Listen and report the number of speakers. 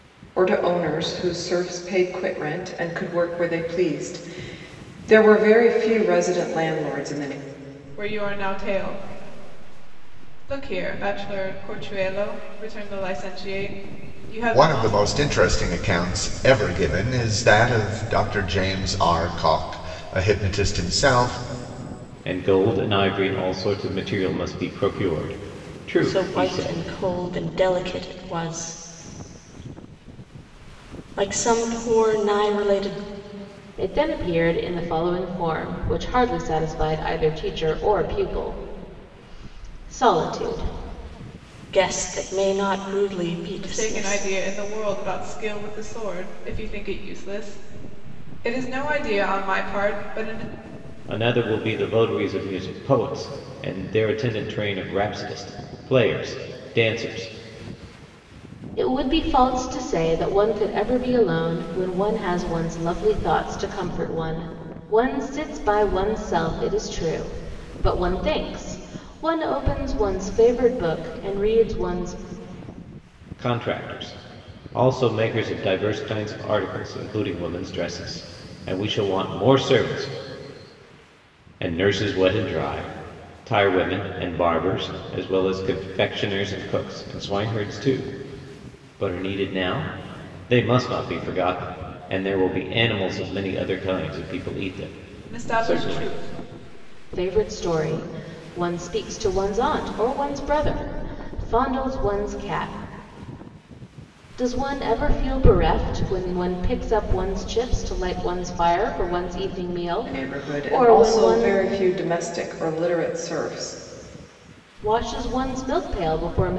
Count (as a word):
six